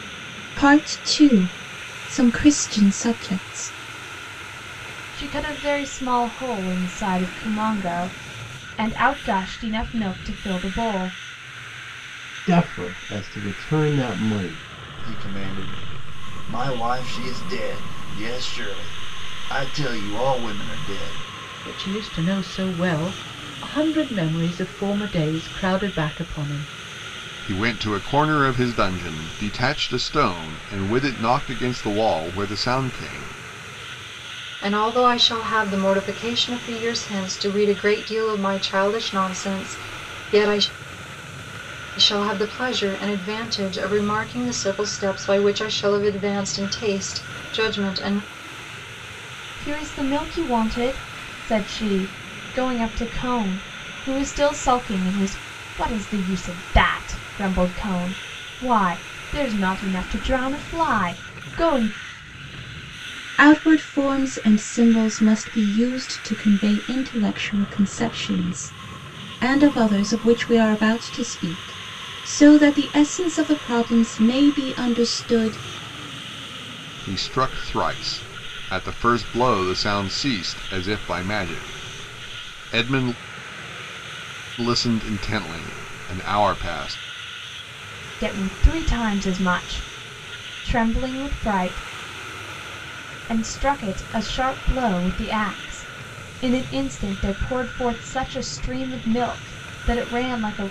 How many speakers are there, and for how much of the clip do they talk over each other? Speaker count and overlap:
seven, no overlap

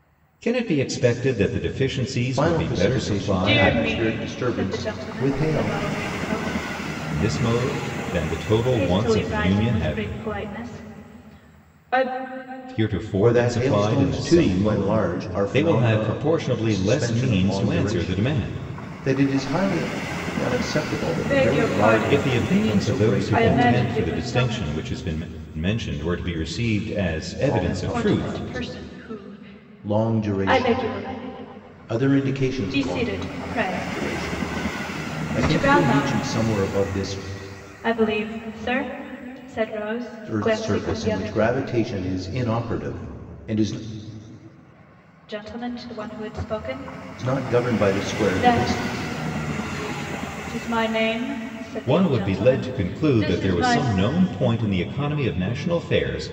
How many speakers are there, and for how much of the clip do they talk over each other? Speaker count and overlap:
three, about 41%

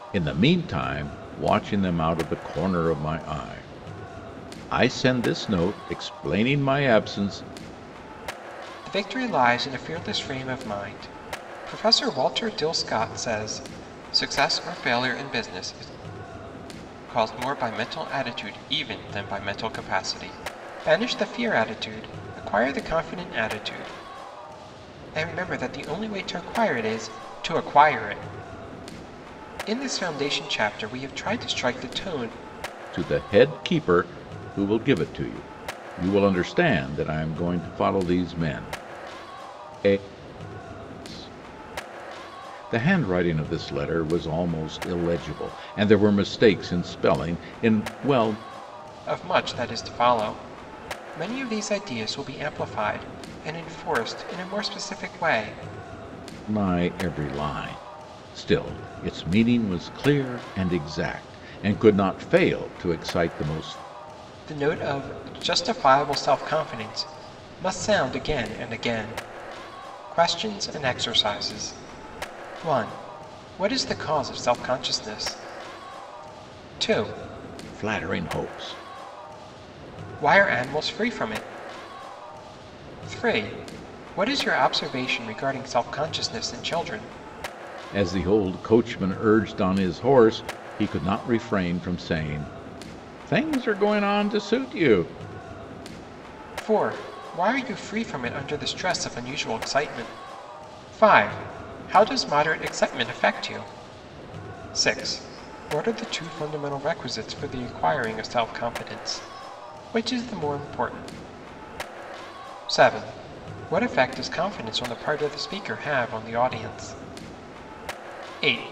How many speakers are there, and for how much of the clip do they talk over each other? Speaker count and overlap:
two, no overlap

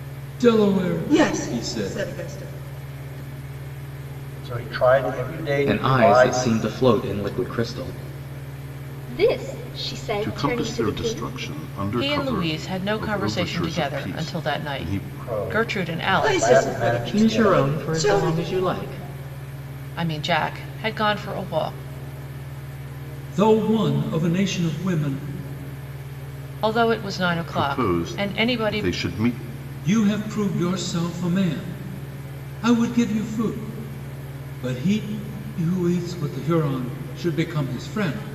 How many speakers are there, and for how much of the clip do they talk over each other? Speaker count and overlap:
seven, about 27%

